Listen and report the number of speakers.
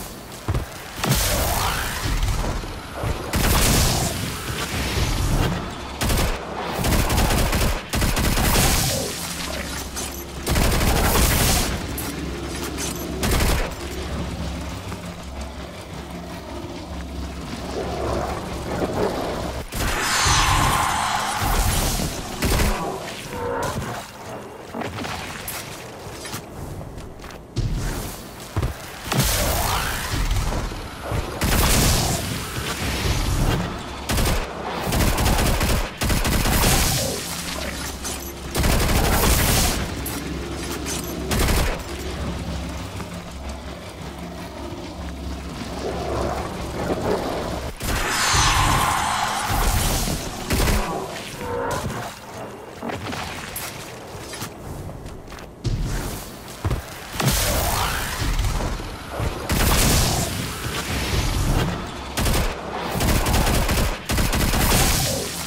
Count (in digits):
0